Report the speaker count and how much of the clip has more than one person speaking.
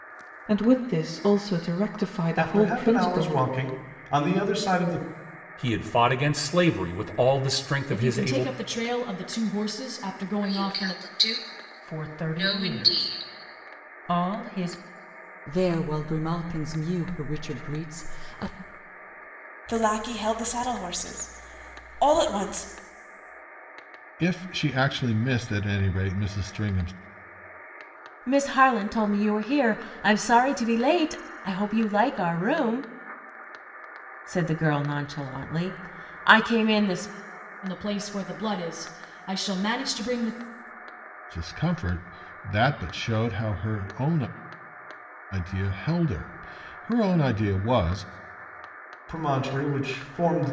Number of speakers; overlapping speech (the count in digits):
10, about 8%